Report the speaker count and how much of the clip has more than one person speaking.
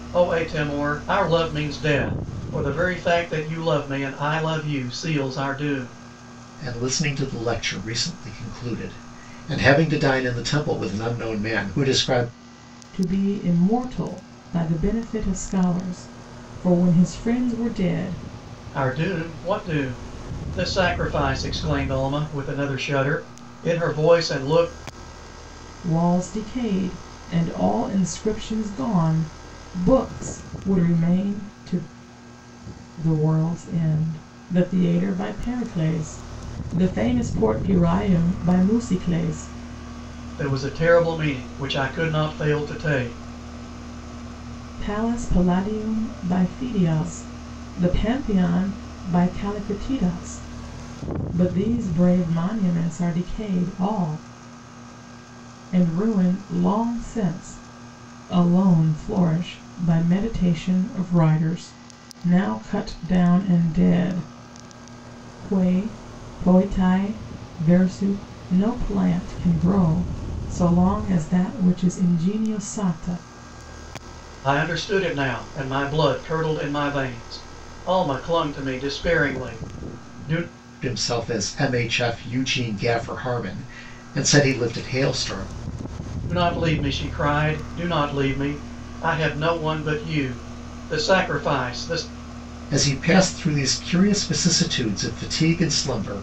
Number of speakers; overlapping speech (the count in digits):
3, no overlap